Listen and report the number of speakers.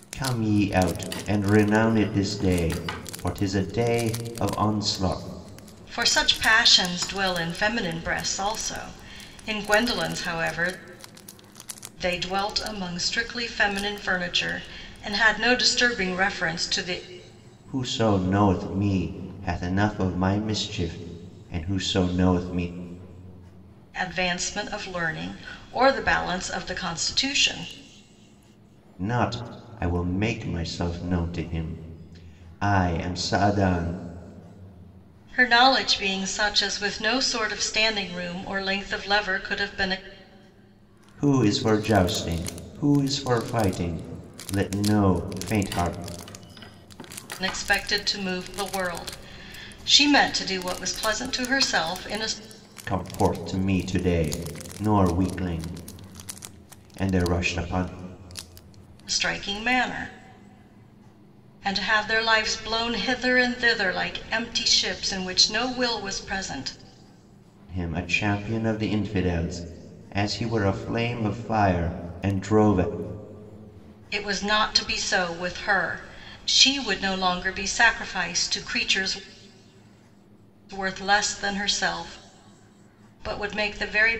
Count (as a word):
two